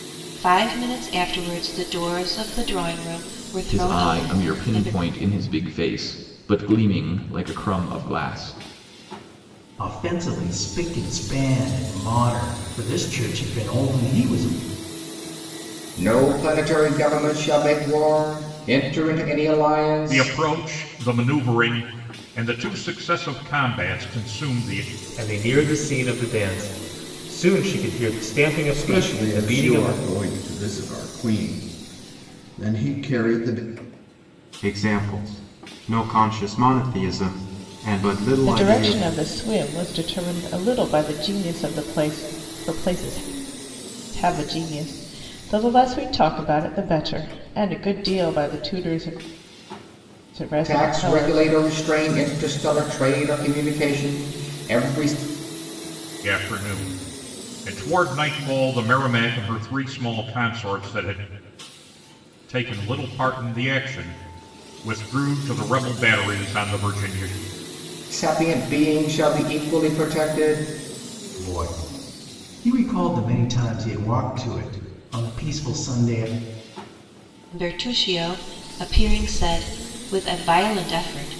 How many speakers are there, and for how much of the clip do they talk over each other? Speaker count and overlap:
nine, about 5%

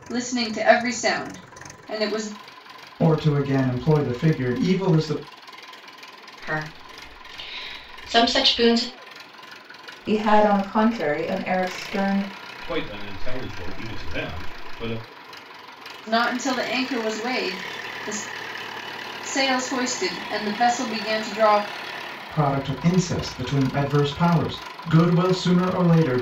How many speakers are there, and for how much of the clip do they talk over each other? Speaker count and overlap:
five, no overlap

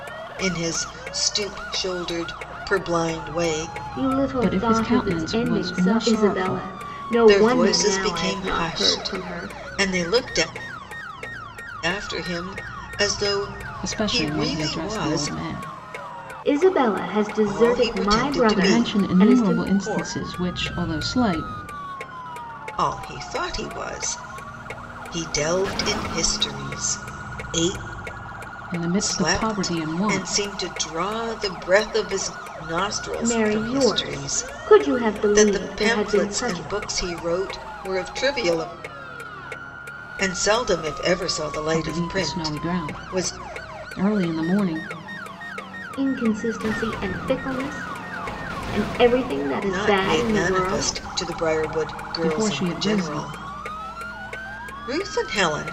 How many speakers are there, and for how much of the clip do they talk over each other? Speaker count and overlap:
three, about 32%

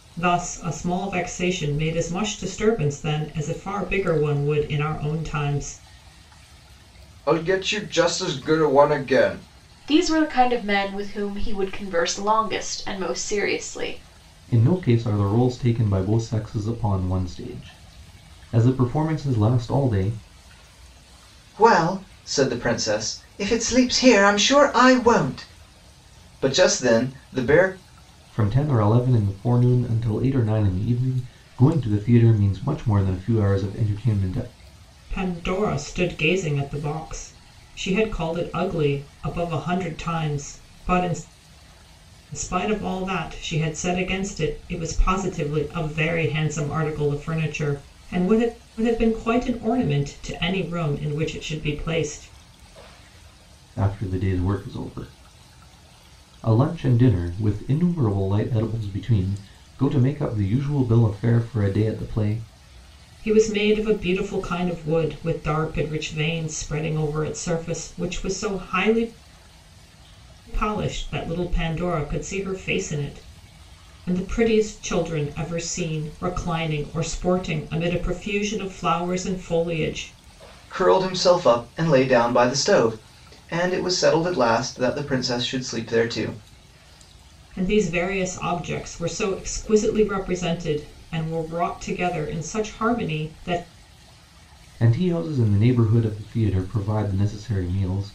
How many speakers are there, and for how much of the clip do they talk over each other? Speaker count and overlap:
four, no overlap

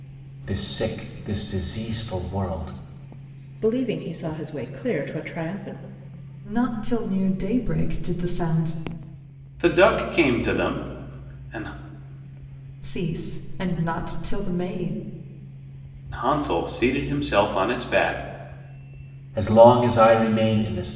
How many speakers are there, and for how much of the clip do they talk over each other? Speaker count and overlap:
four, no overlap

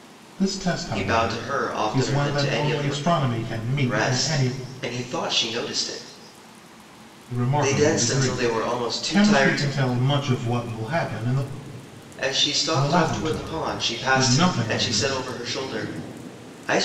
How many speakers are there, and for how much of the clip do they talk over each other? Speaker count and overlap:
two, about 41%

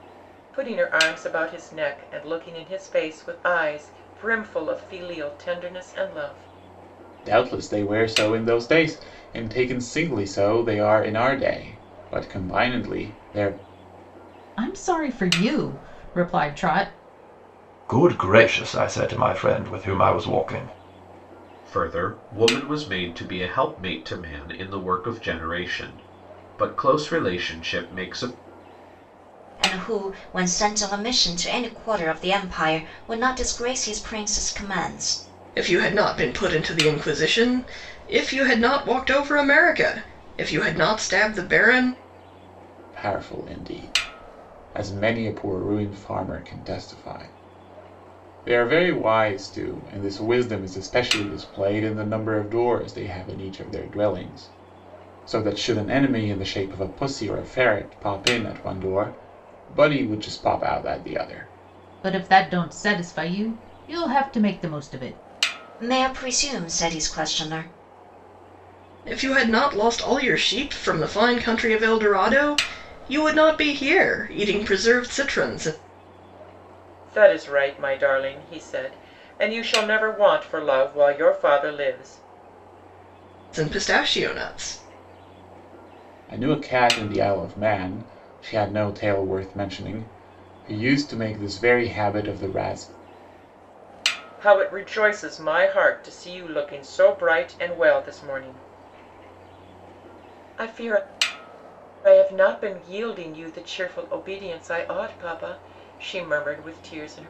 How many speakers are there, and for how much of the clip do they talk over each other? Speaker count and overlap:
seven, no overlap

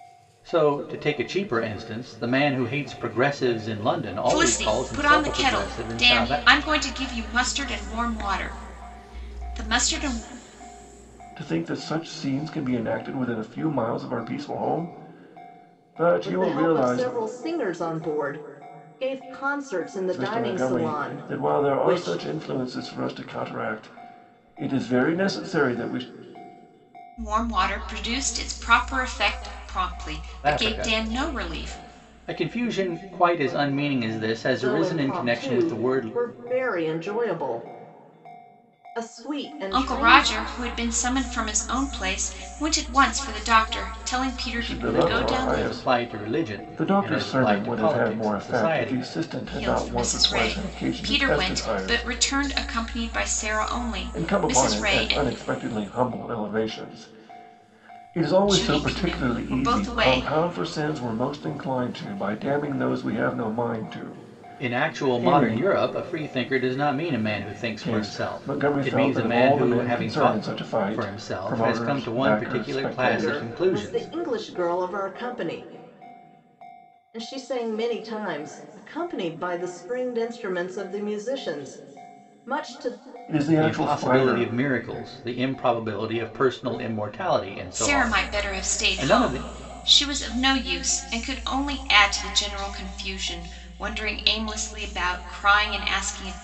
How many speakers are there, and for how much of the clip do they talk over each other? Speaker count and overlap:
four, about 29%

